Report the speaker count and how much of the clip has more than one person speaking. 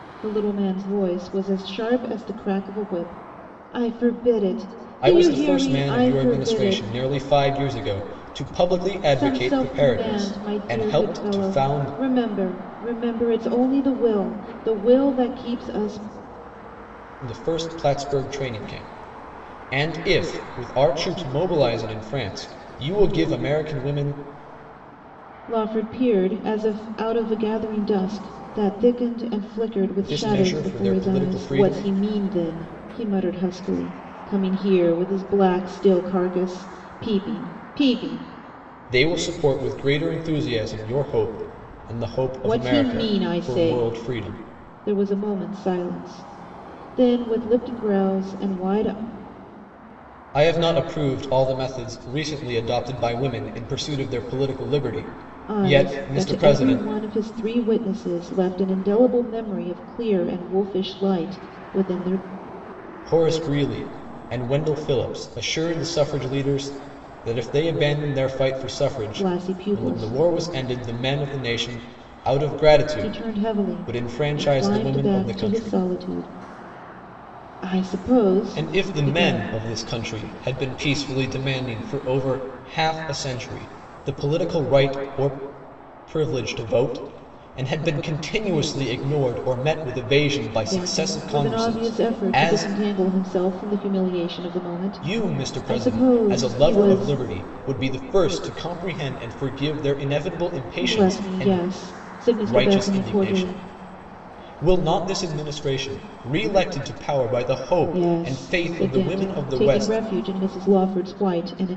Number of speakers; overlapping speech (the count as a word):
two, about 21%